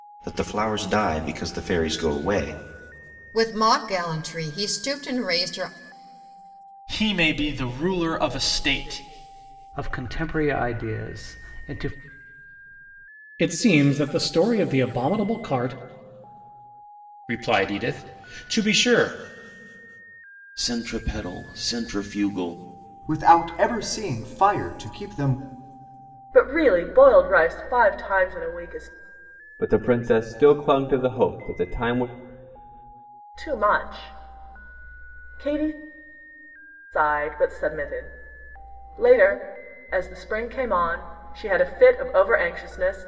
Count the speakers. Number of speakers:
10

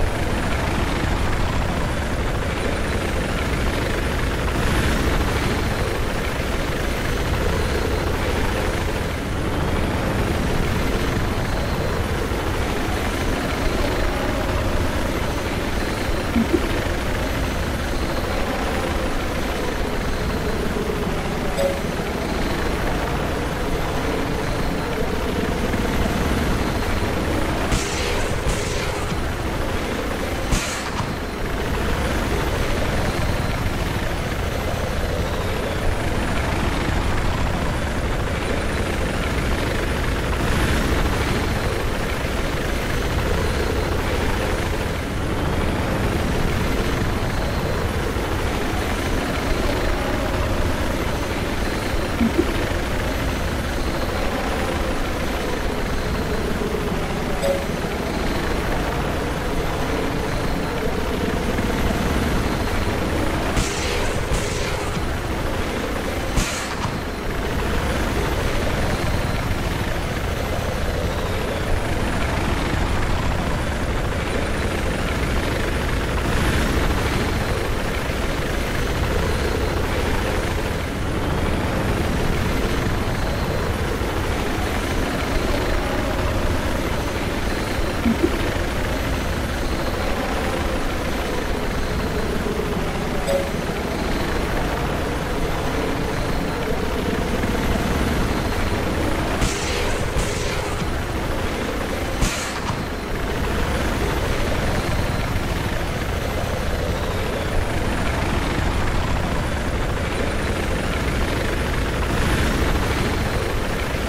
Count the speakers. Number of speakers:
0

